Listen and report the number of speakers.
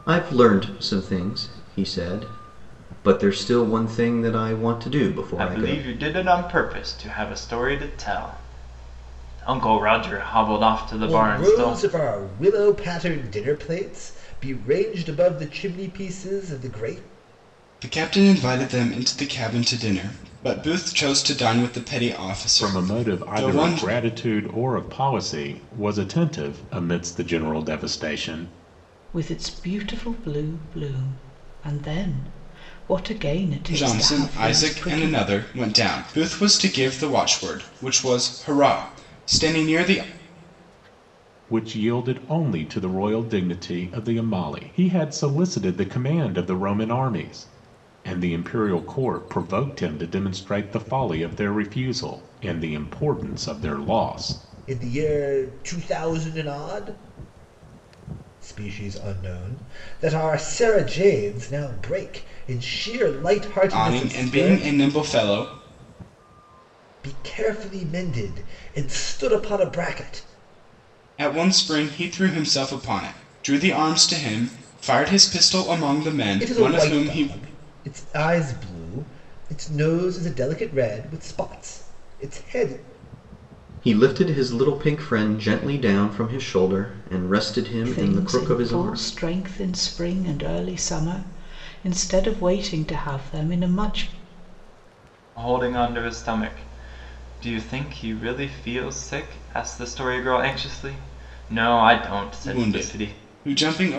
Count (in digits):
6